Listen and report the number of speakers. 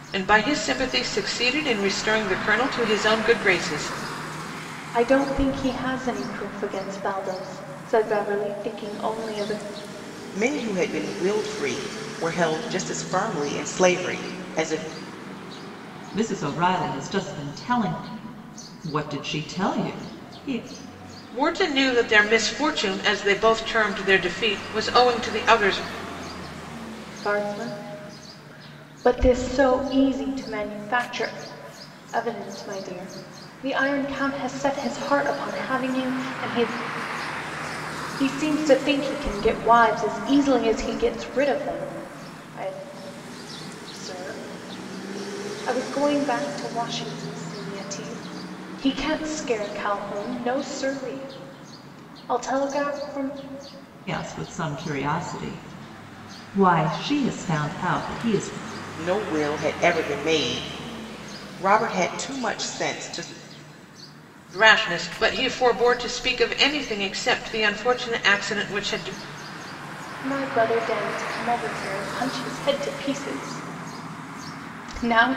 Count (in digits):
4